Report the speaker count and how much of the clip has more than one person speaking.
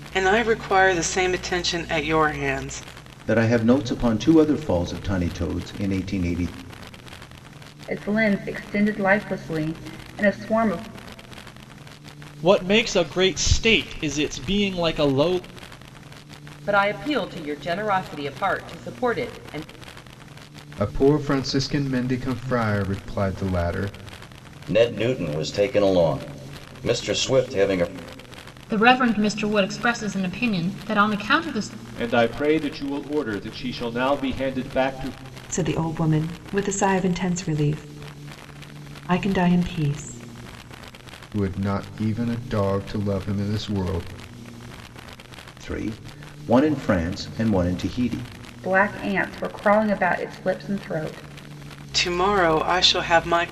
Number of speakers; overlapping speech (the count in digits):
10, no overlap